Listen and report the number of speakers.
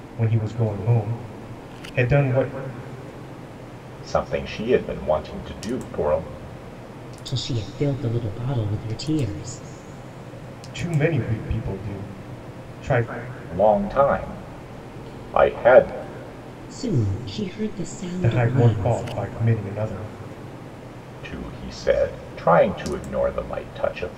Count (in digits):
3